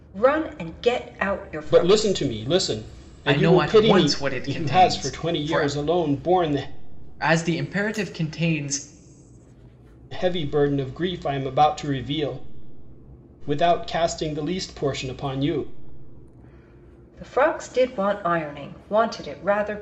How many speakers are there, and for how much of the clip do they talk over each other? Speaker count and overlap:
3, about 13%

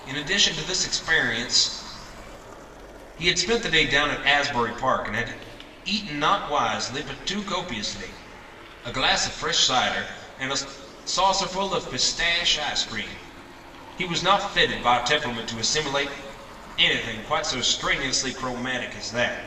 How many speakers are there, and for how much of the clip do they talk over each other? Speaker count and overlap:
1, no overlap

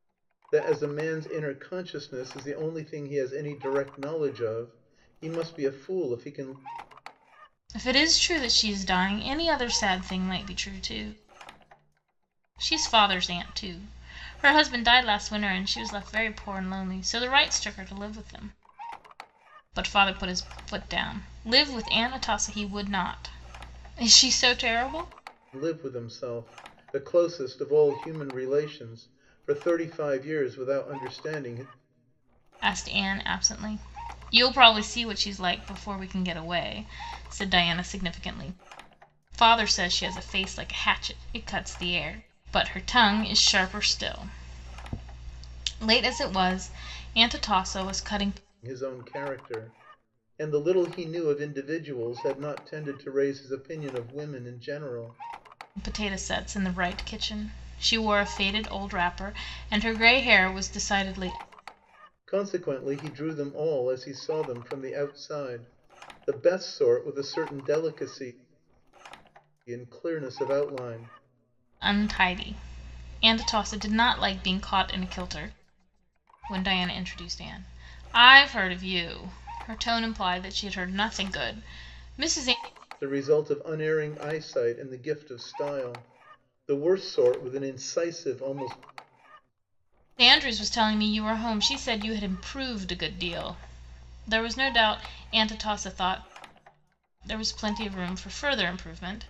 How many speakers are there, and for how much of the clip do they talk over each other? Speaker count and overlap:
2, no overlap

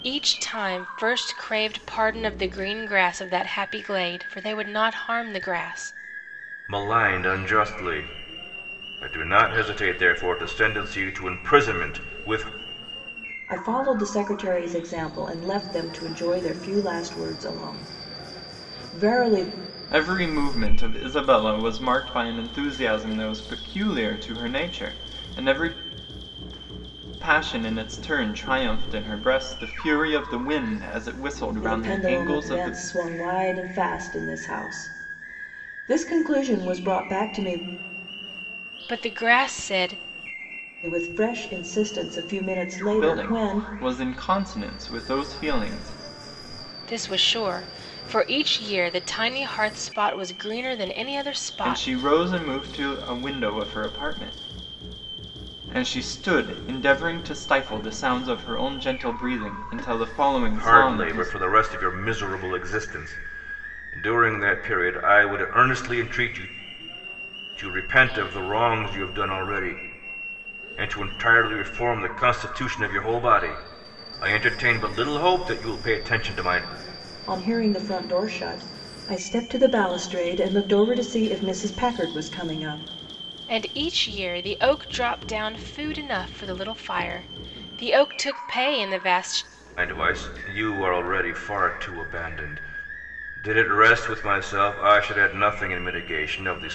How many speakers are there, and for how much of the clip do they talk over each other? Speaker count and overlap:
4, about 3%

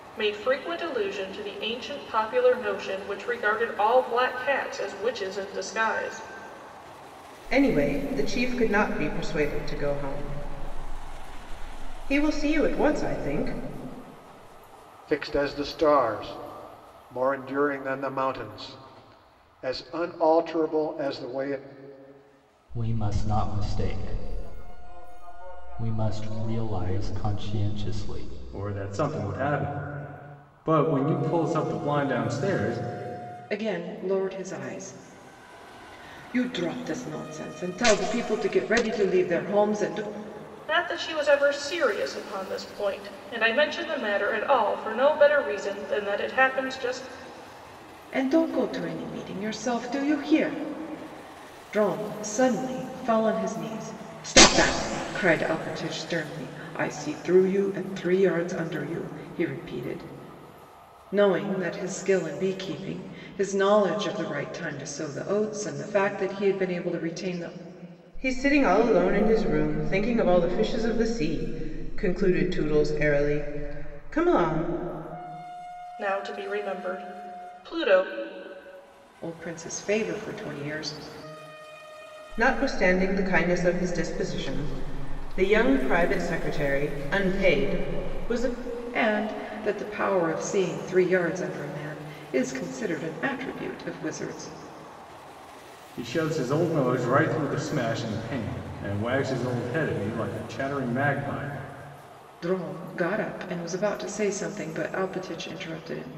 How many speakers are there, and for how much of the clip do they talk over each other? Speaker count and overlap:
6, no overlap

